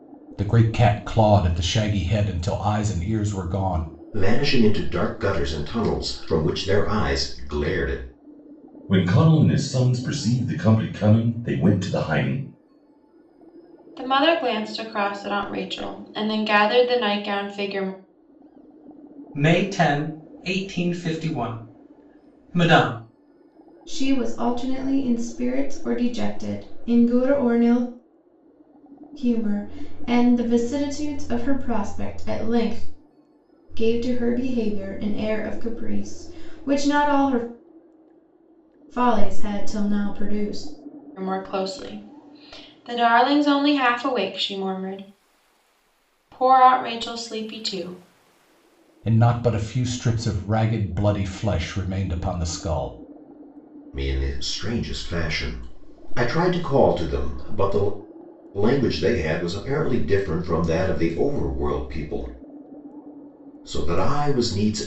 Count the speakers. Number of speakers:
6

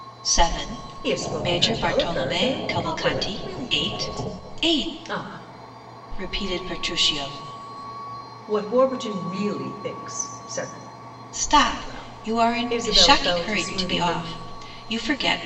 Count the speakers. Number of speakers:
2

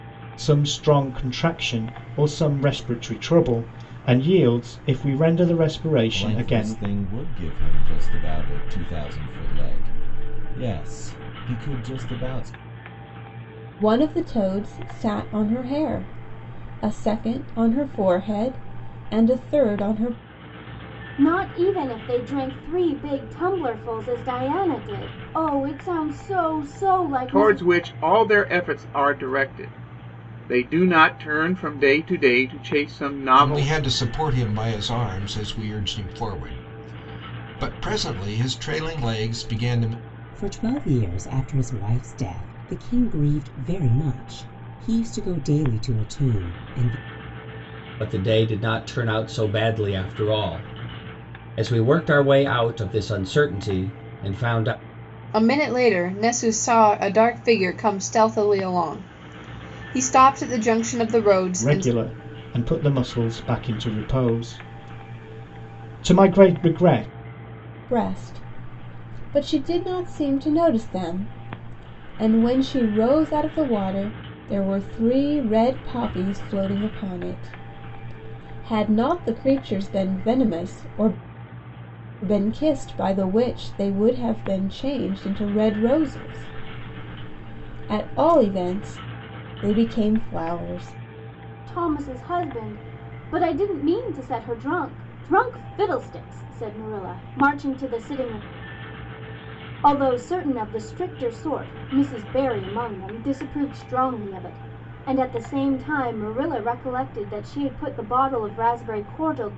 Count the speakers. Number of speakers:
9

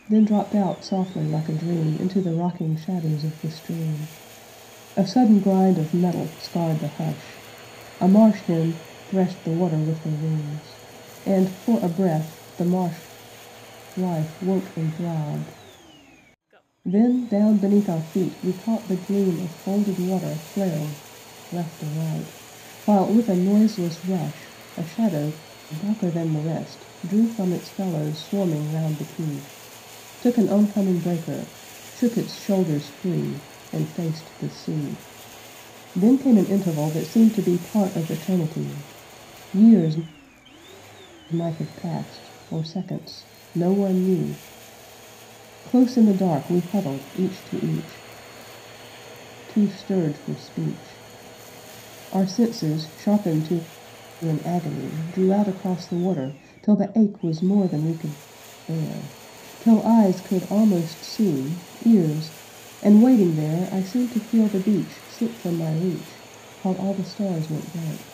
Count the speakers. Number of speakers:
1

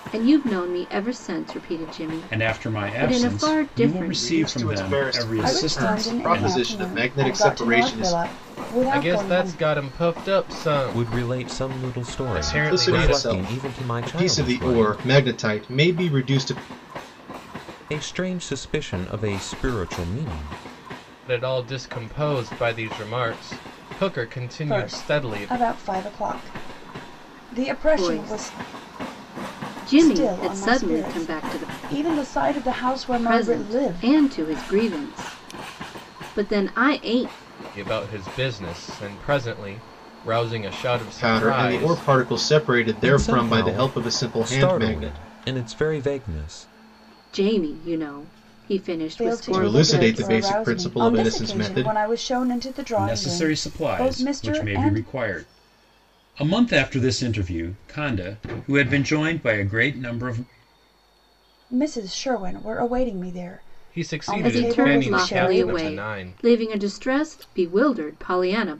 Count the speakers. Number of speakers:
6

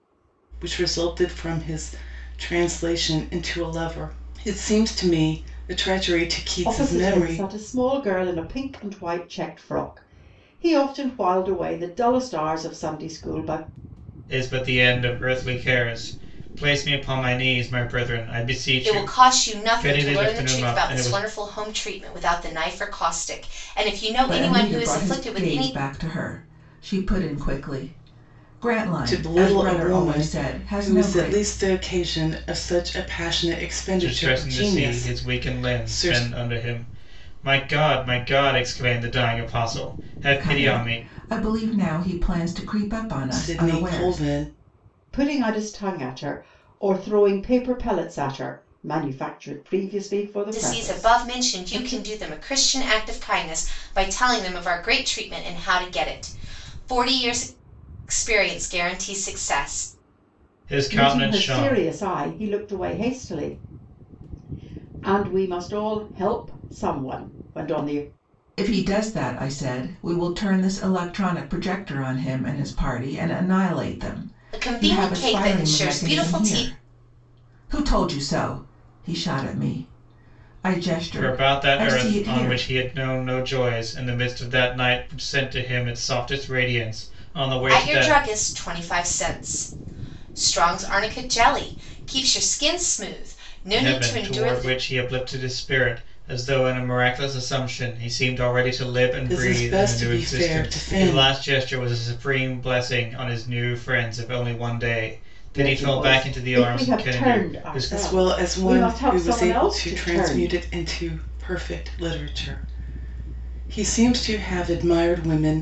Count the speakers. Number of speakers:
5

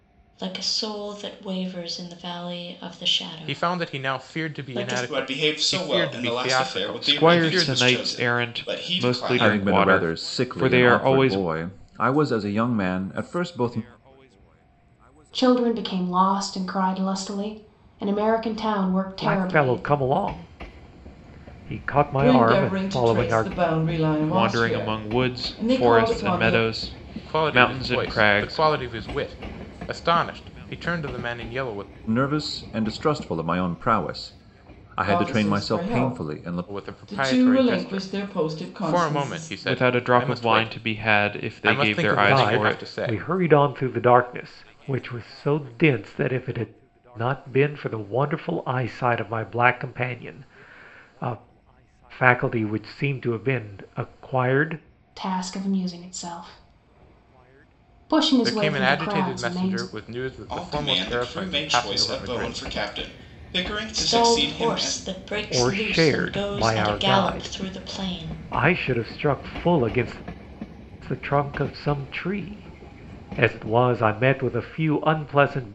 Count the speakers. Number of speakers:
8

